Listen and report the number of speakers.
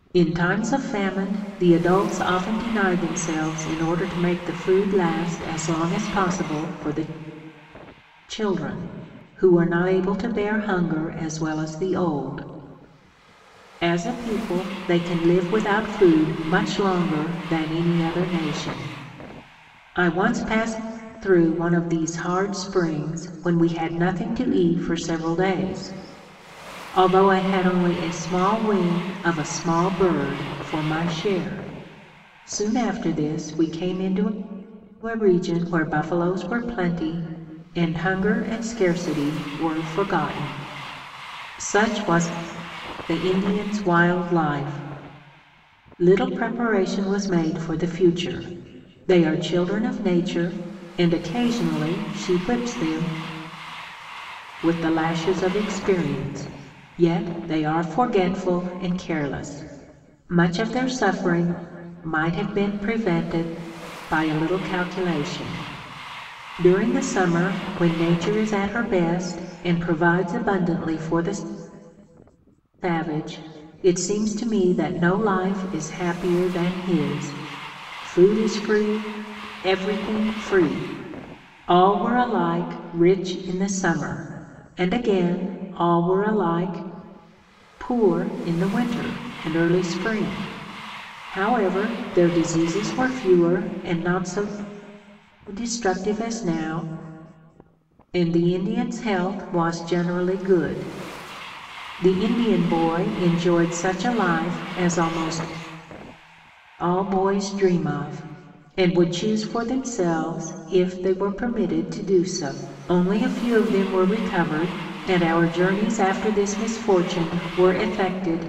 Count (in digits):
1